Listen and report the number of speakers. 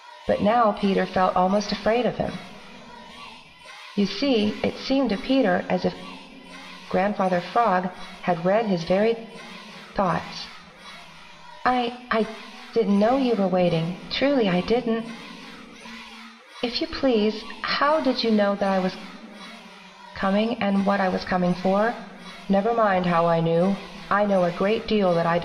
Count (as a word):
one